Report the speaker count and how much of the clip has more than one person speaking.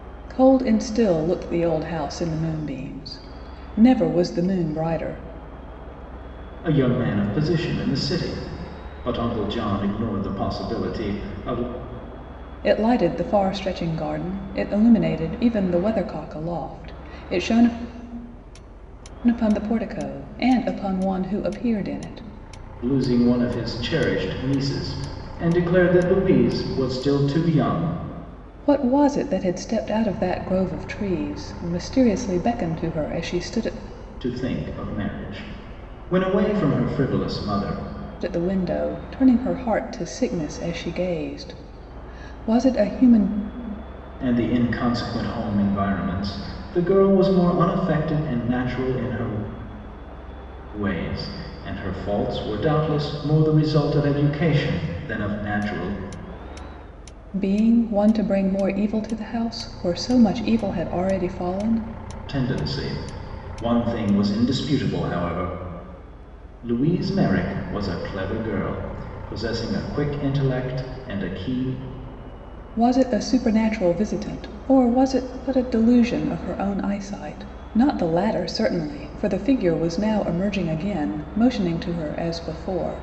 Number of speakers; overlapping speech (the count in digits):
2, no overlap